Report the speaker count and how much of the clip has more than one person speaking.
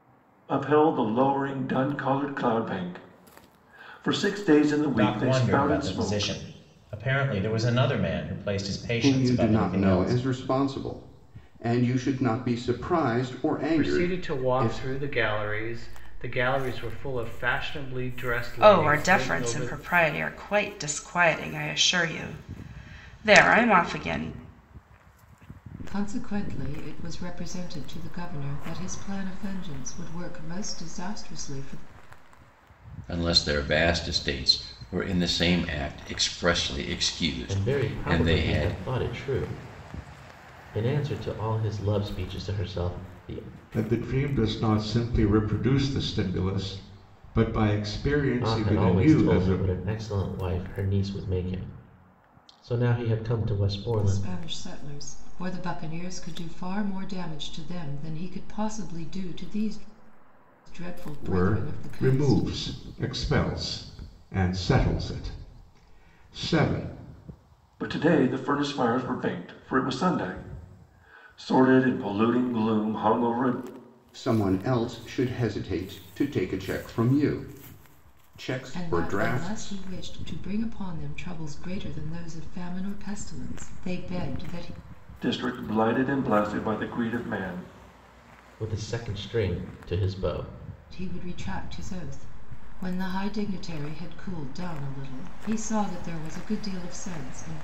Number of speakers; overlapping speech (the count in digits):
9, about 11%